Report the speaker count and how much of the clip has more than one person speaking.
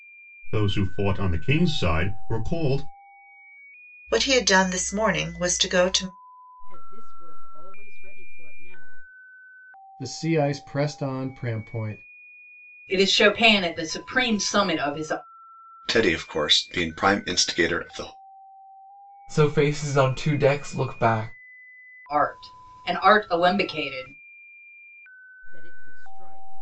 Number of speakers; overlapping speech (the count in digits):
7, no overlap